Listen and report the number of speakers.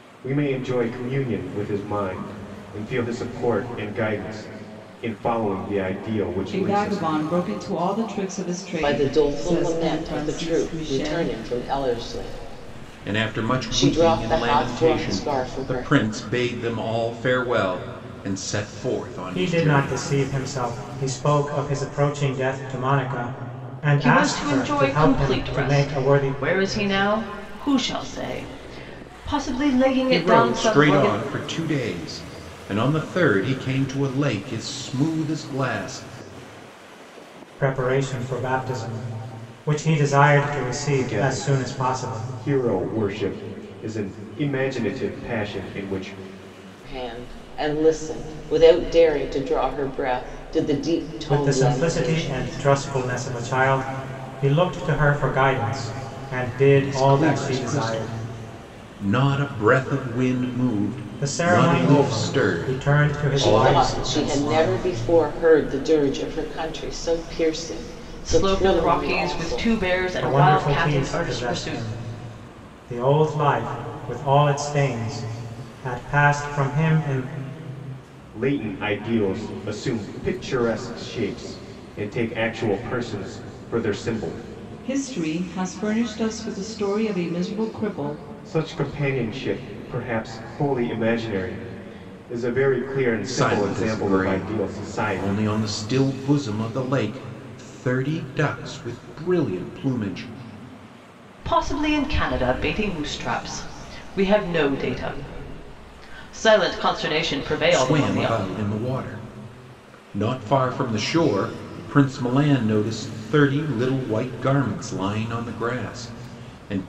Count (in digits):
6